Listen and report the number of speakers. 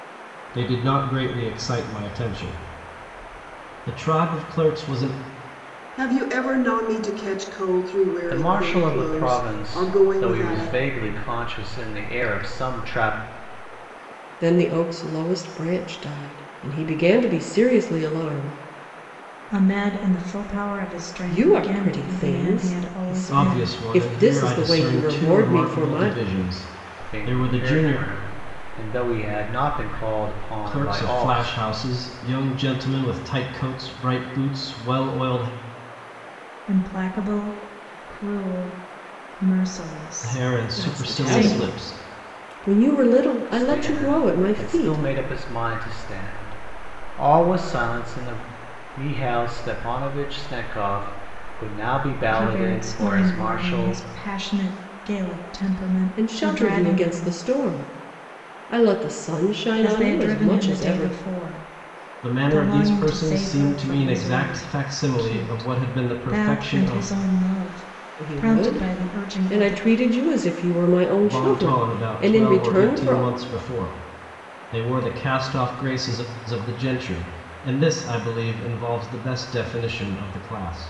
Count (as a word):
five